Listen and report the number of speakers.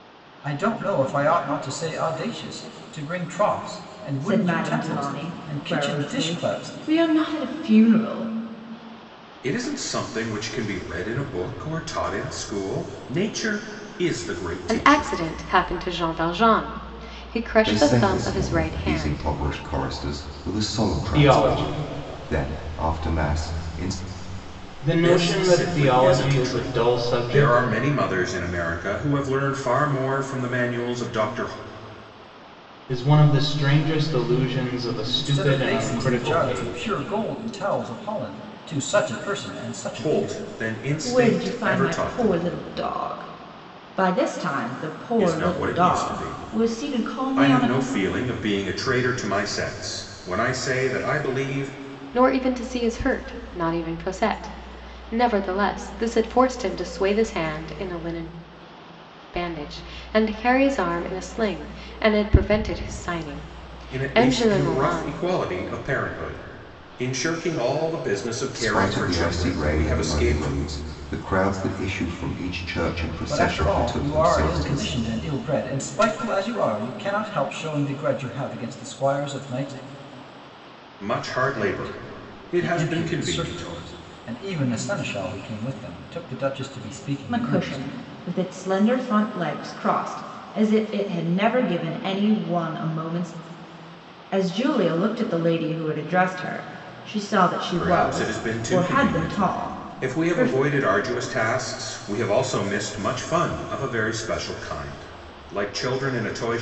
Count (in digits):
6